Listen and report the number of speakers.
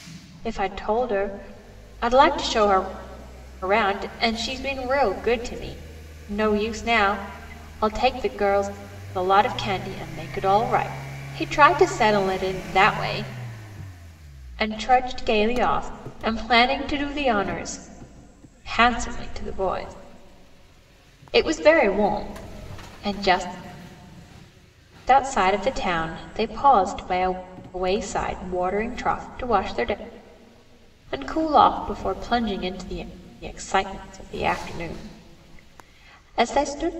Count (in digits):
1